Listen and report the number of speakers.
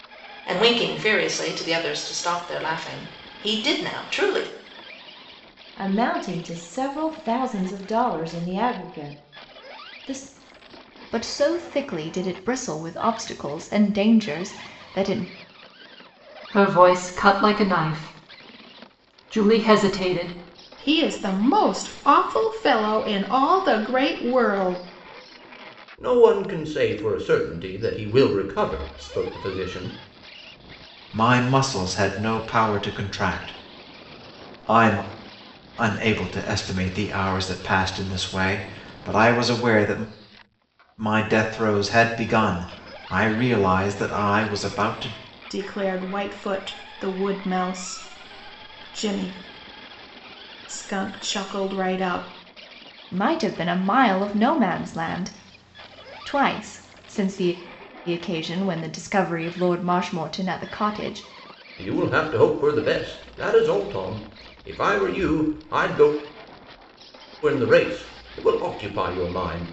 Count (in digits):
7